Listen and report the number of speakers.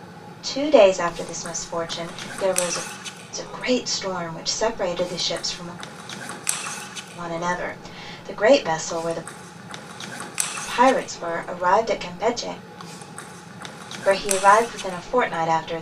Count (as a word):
one